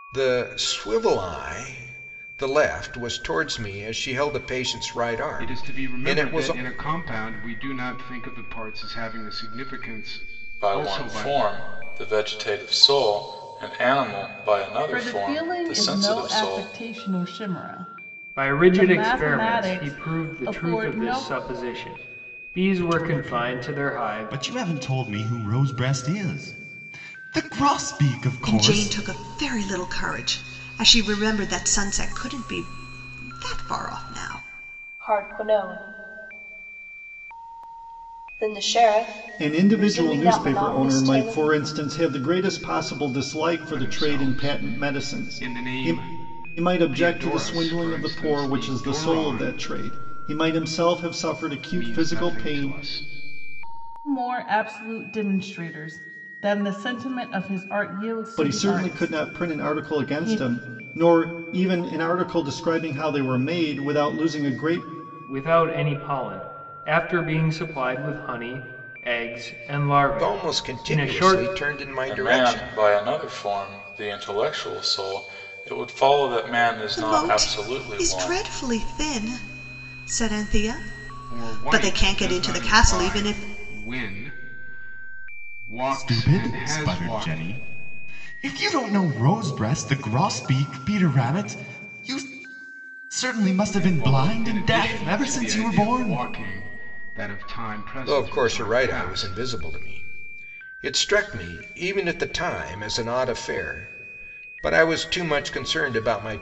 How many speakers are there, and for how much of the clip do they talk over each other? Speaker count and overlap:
nine, about 29%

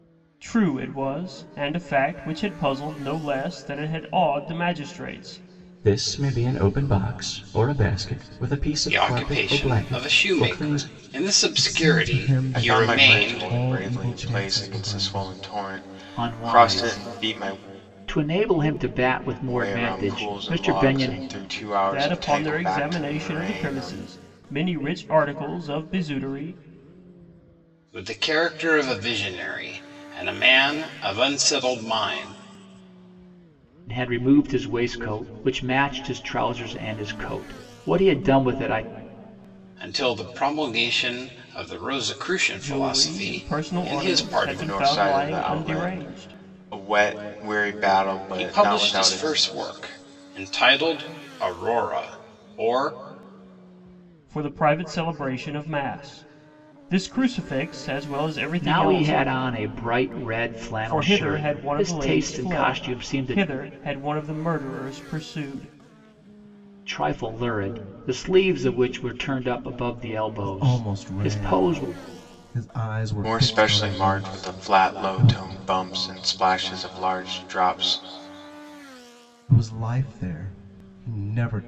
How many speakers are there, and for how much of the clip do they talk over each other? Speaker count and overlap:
six, about 28%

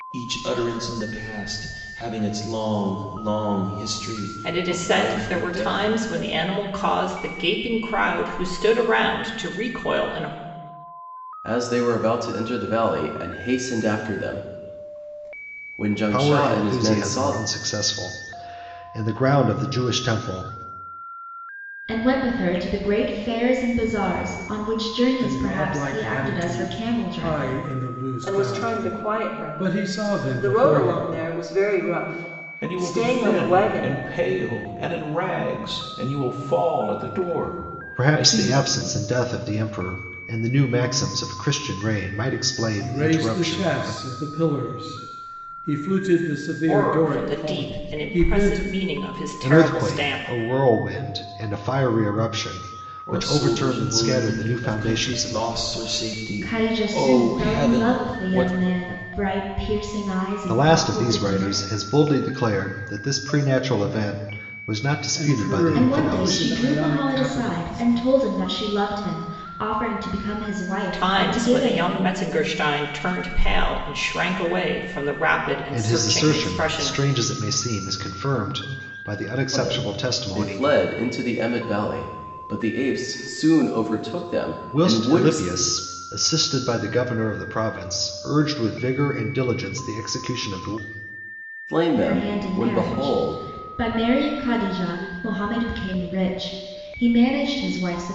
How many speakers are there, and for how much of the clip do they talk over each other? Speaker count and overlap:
eight, about 29%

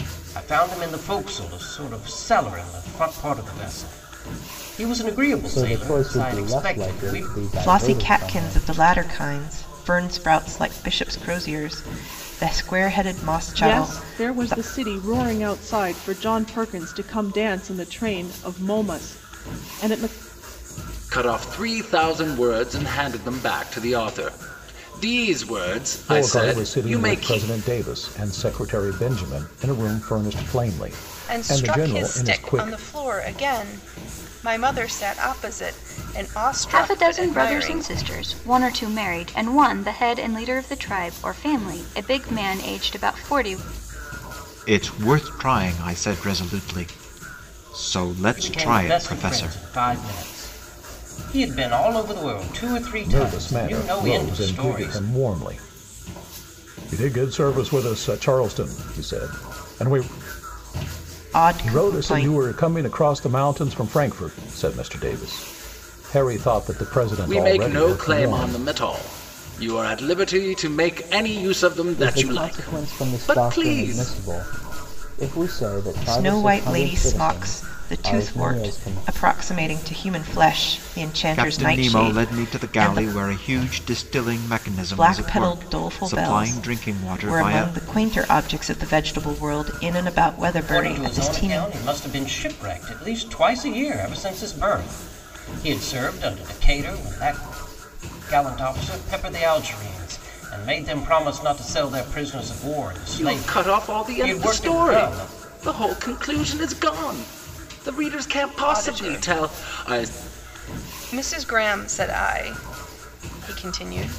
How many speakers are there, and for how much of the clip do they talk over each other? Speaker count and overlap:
nine, about 25%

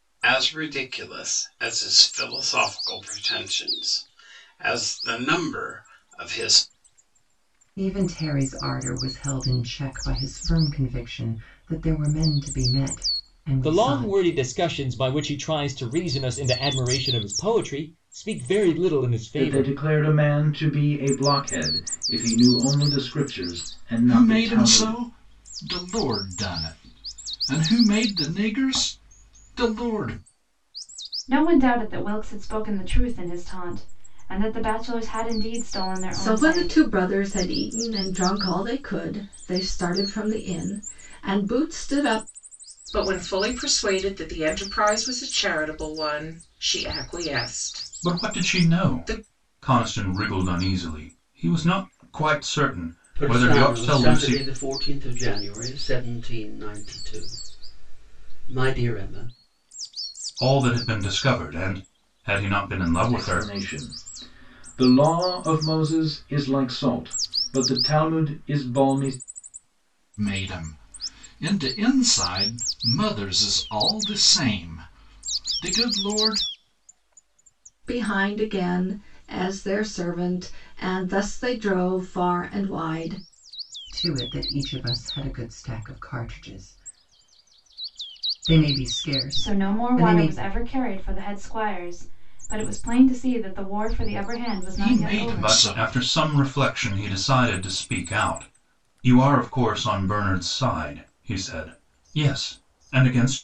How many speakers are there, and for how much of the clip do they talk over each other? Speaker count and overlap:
ten, about 7%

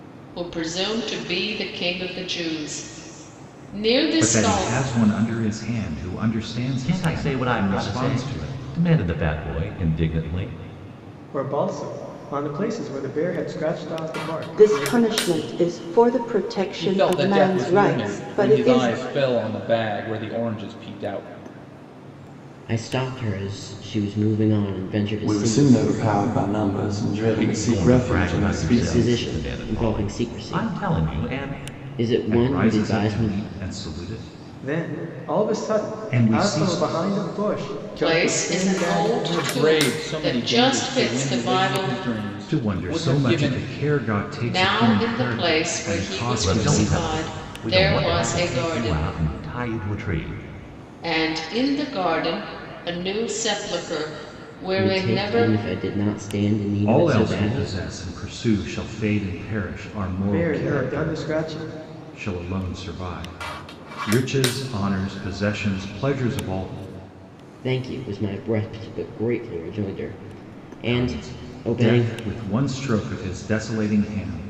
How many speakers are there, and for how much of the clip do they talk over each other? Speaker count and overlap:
eight, about 38%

